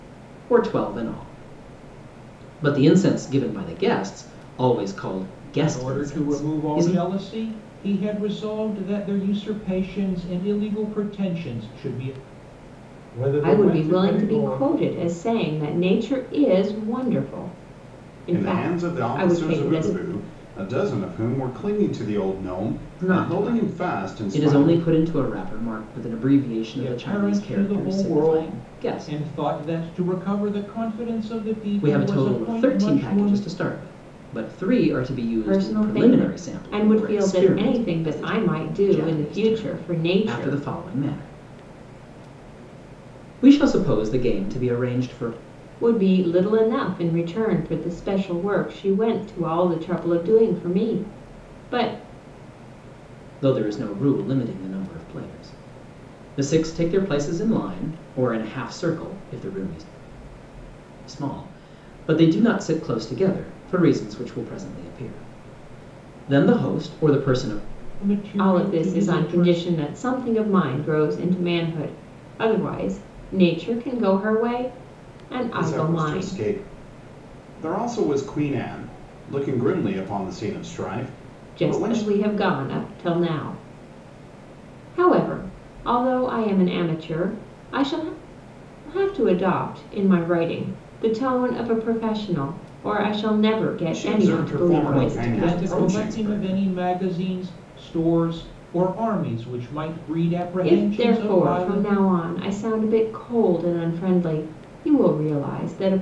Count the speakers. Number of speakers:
four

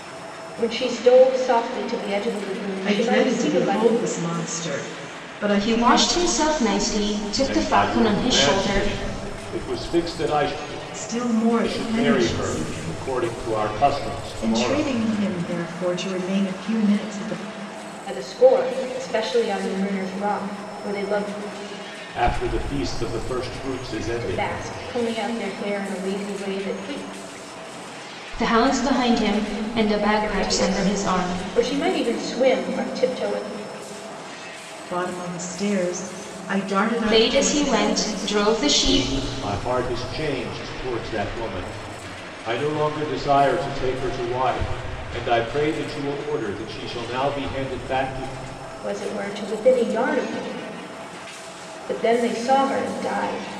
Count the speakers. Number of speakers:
four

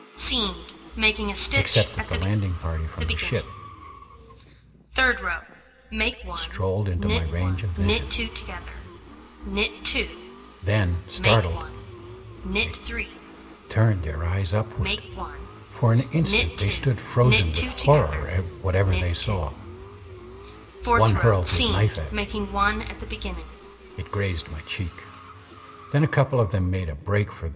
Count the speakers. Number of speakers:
two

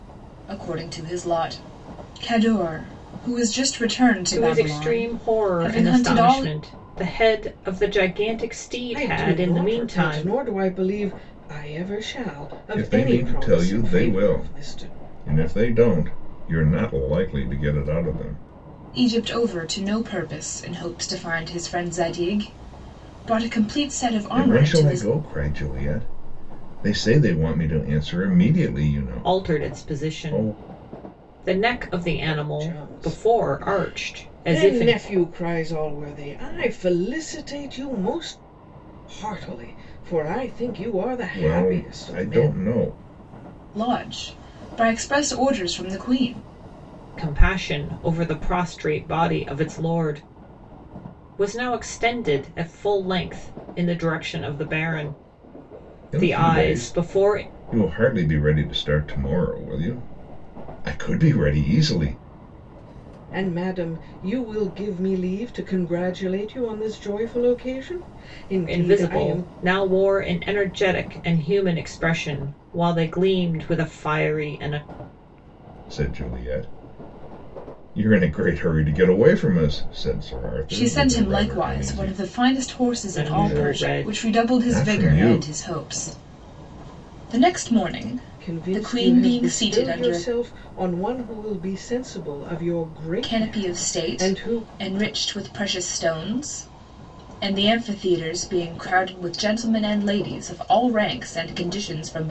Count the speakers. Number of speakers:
four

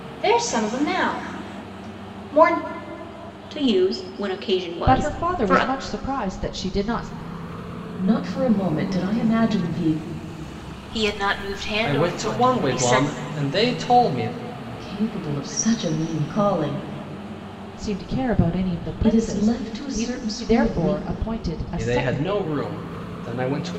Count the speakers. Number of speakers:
six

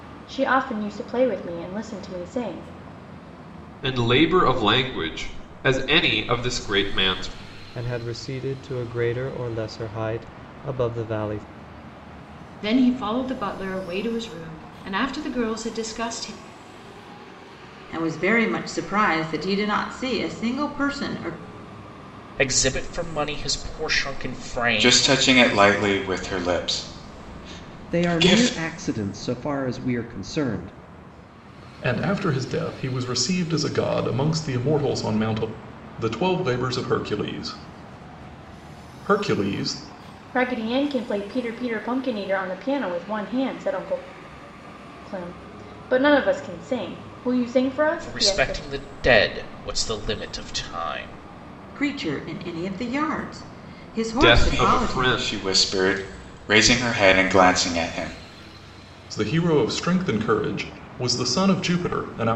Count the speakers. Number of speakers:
nine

